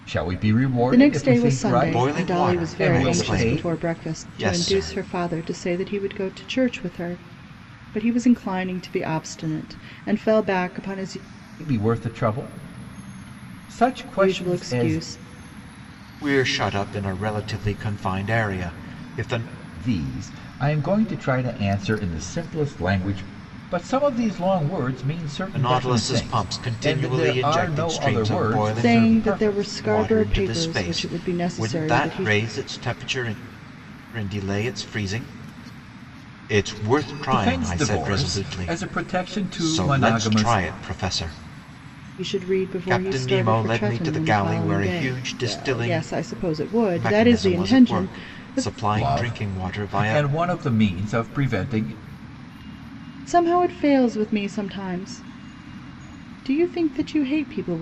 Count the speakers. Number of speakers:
3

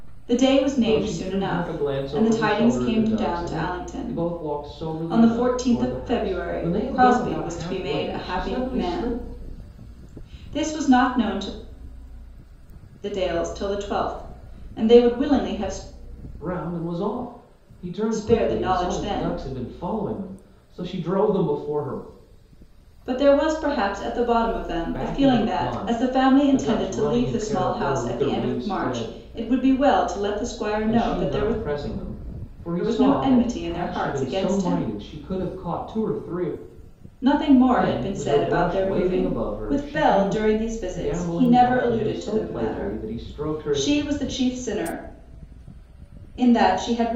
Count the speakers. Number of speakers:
2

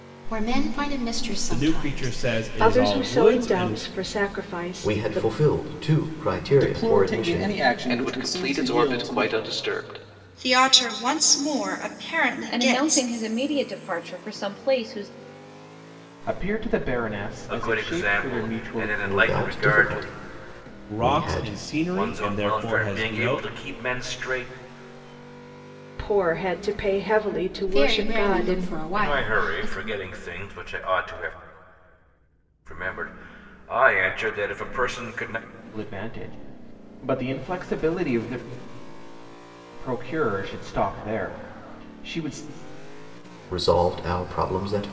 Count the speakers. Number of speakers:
10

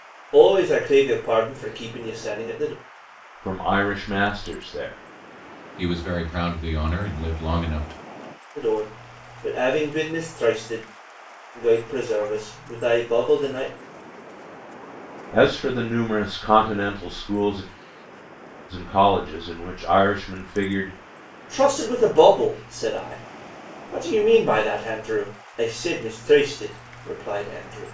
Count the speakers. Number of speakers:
3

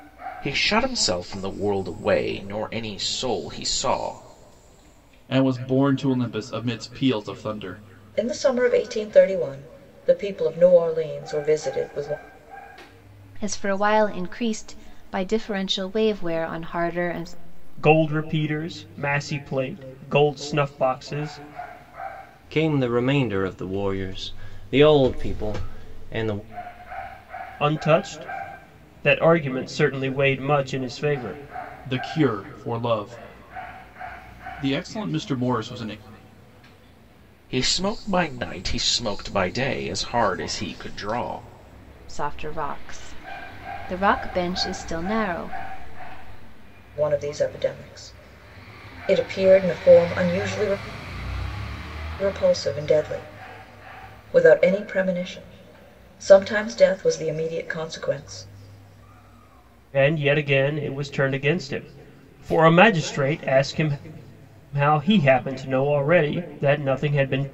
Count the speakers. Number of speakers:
6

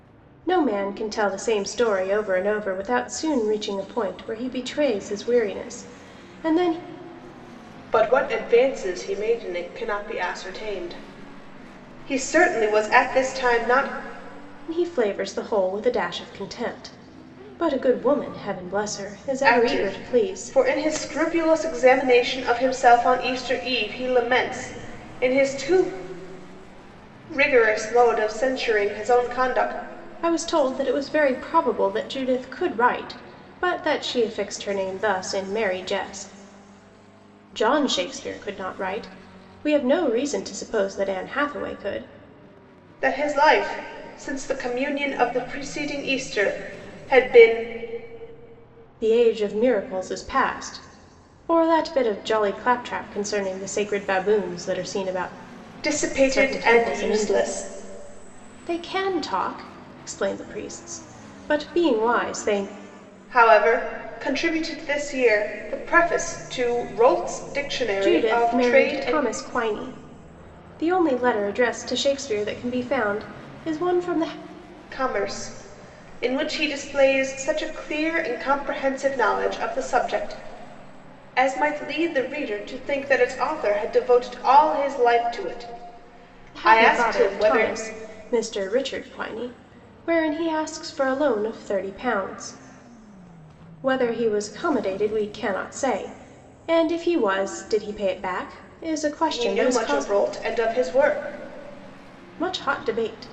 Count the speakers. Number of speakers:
2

